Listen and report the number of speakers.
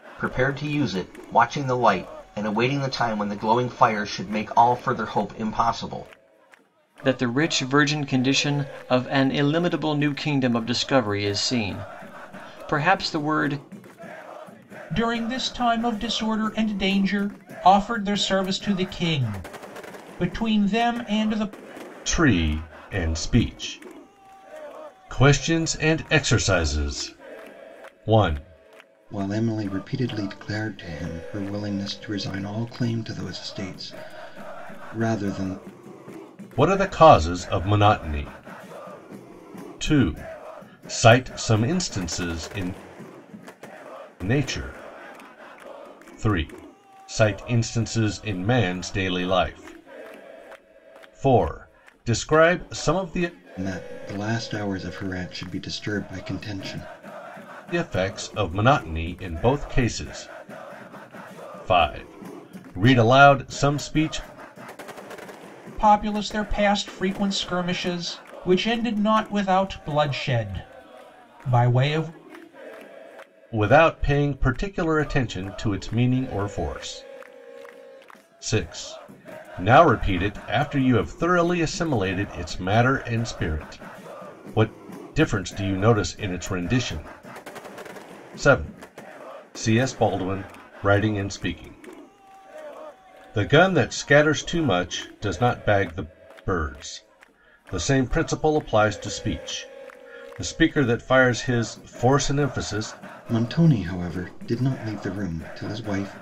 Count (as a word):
five